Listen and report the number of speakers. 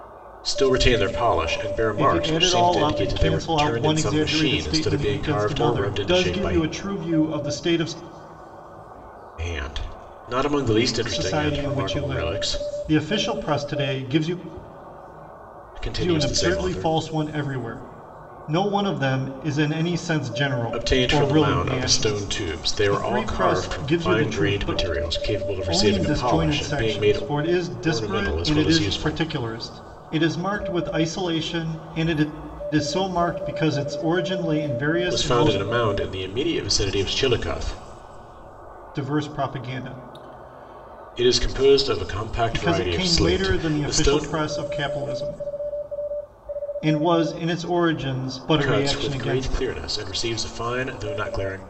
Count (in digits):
2